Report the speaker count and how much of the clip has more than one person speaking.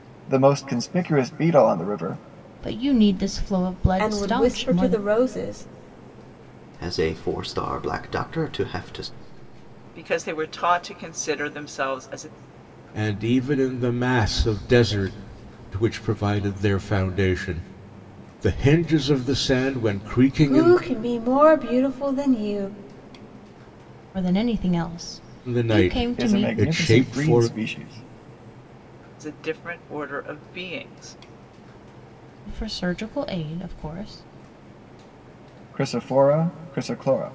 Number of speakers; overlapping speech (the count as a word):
six, about 9%